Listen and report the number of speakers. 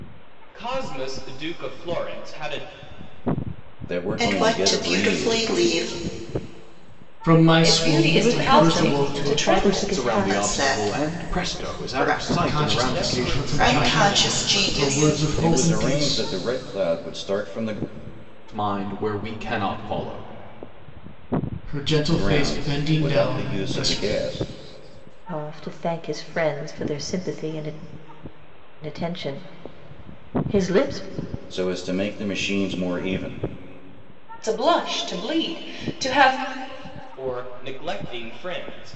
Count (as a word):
seven